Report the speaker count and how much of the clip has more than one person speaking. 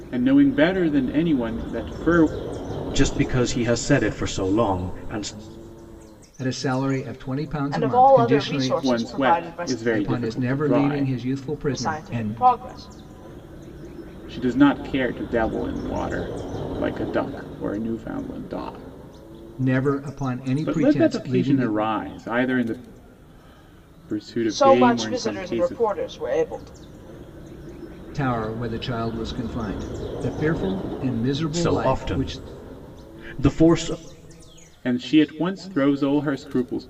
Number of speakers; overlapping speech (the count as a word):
four, about 20%